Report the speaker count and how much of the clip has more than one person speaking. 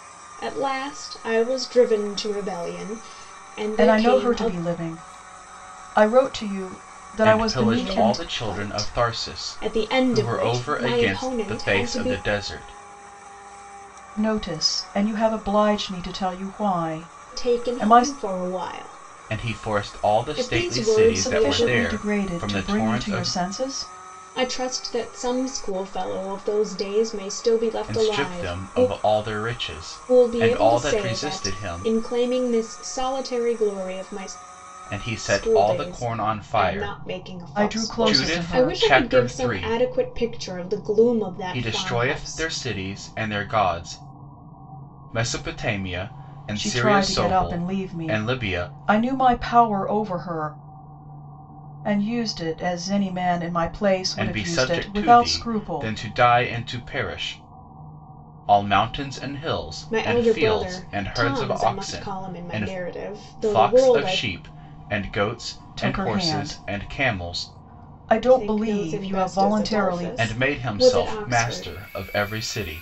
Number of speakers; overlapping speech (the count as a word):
three, about 43%